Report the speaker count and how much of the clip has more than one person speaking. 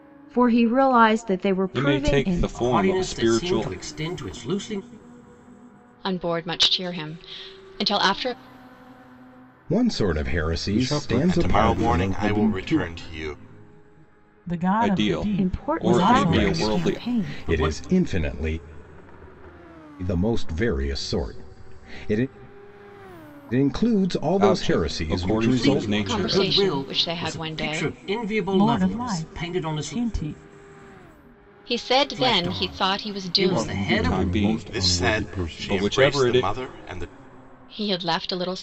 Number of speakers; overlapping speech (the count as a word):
eight, about 43%